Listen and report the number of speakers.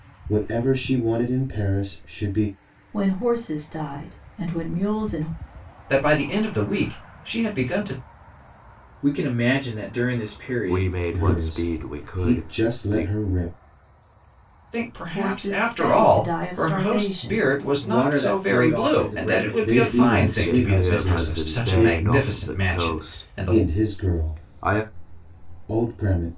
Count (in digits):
5